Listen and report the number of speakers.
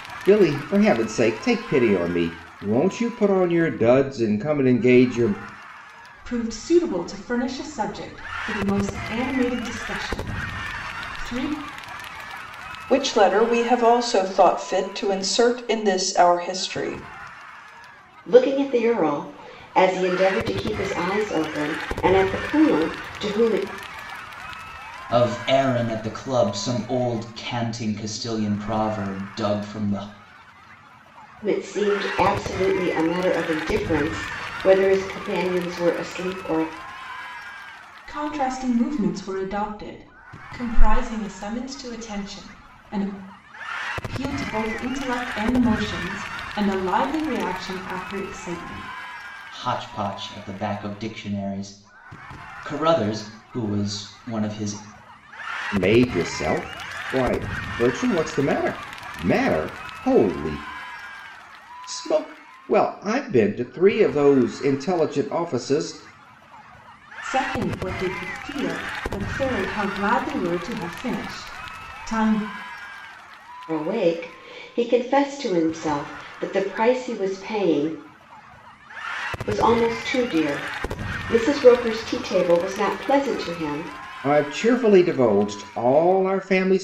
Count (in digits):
5